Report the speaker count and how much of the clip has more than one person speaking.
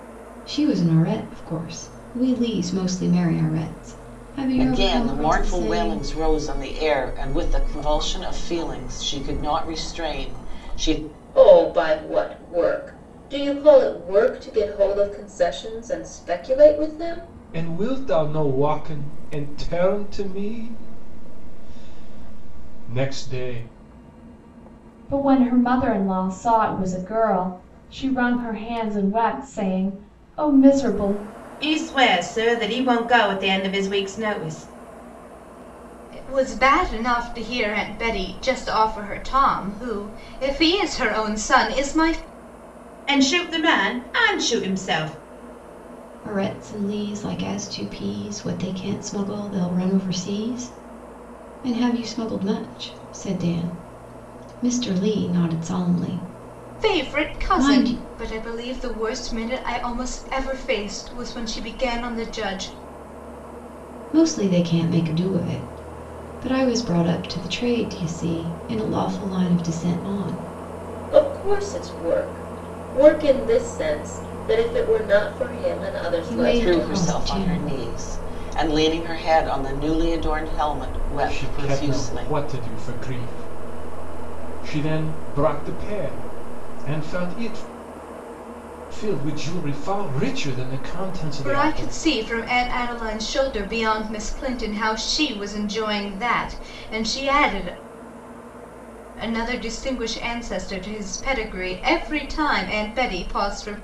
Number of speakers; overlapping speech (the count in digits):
7, about 6%